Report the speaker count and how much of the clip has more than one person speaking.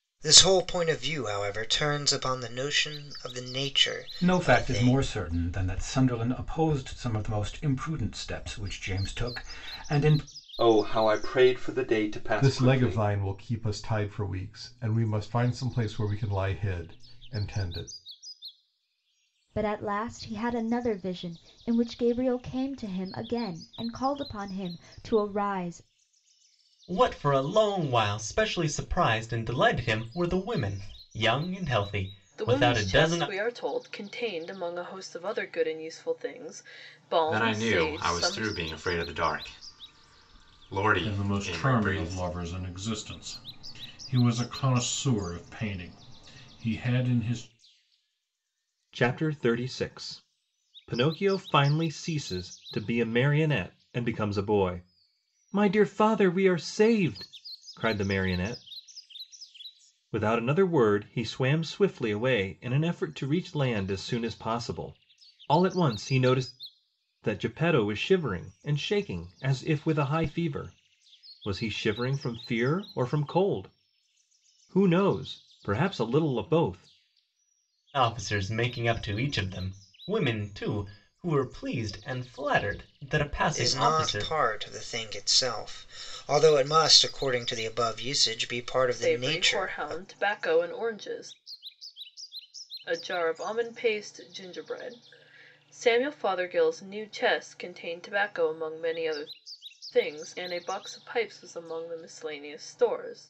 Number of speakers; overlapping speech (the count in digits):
10, about 7%